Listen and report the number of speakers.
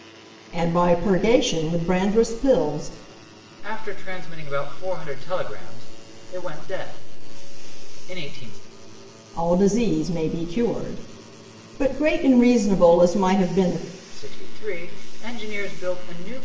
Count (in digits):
2